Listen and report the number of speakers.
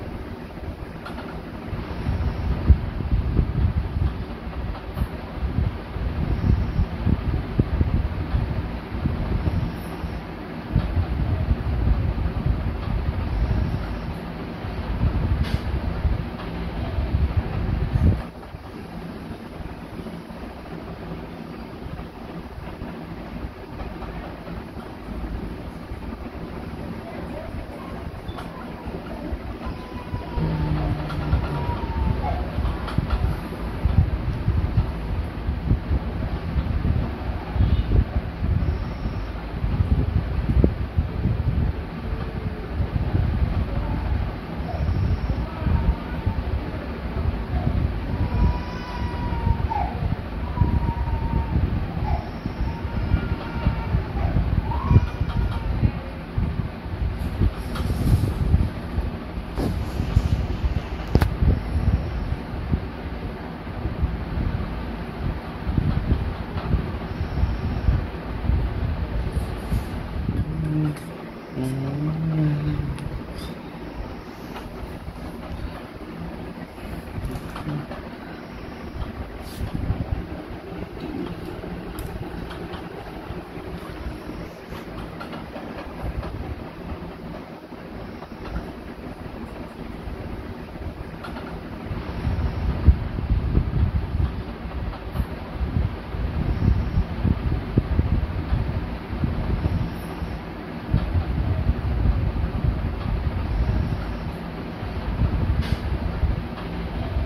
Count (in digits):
0